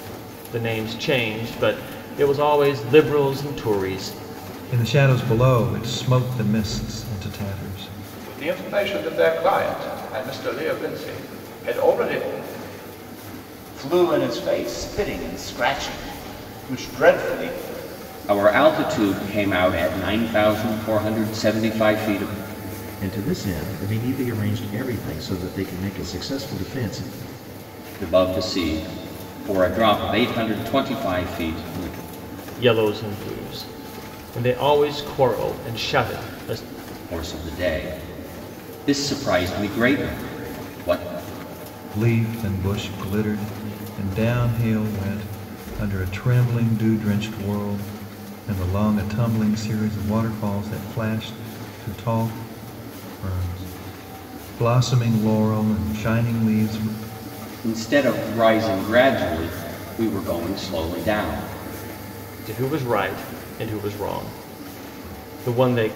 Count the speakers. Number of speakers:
6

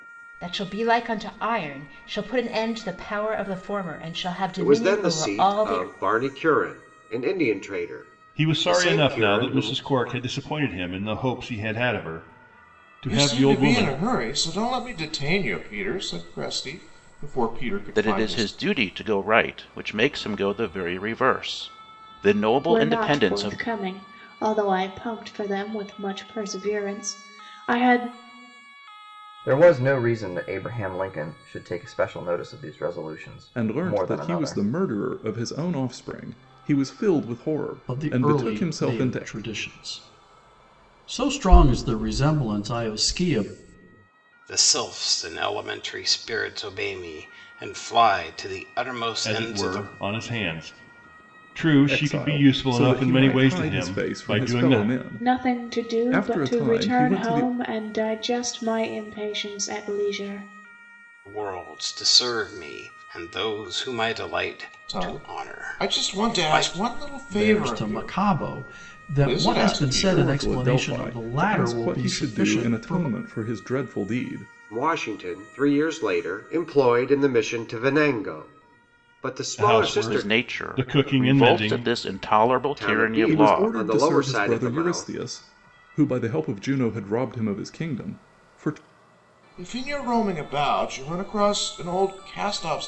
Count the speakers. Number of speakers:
10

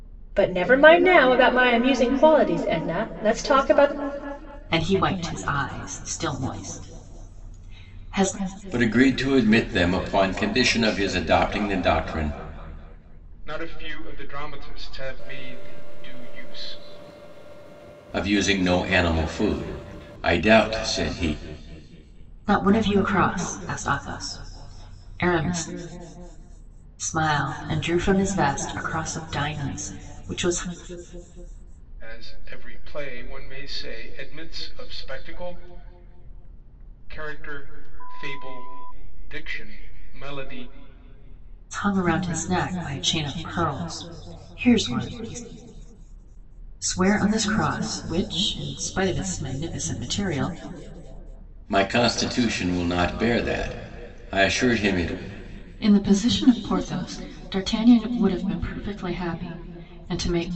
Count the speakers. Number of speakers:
4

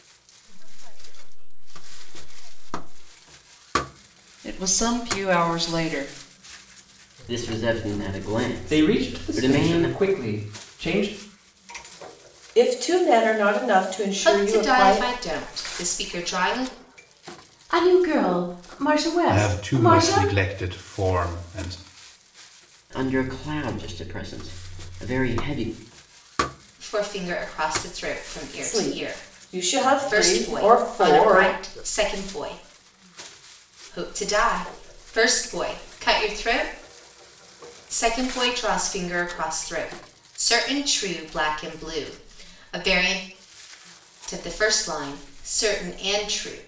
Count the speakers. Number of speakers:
8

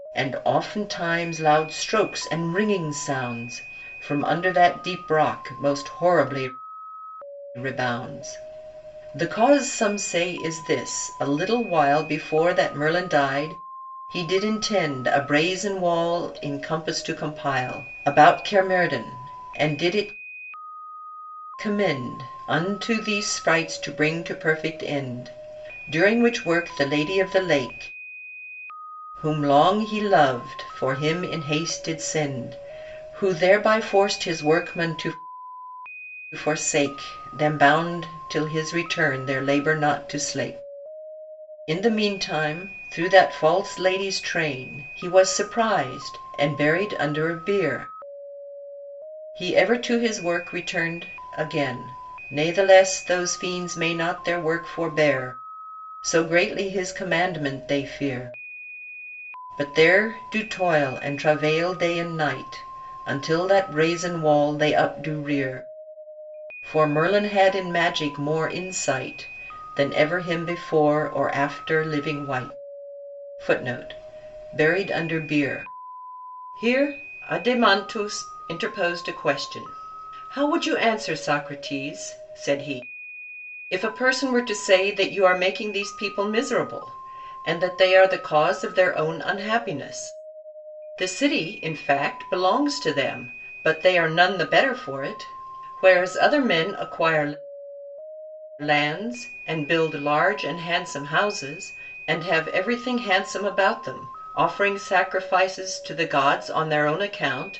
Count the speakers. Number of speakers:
1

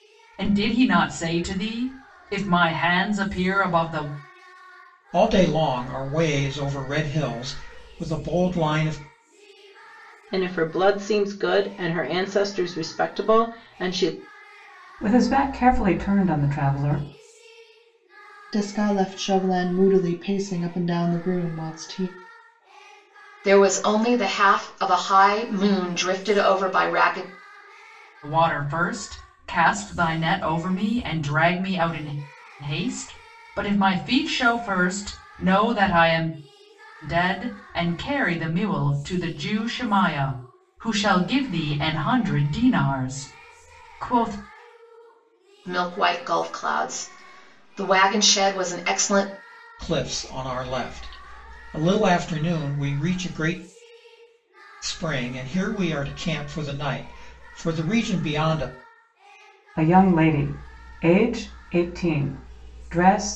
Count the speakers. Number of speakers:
6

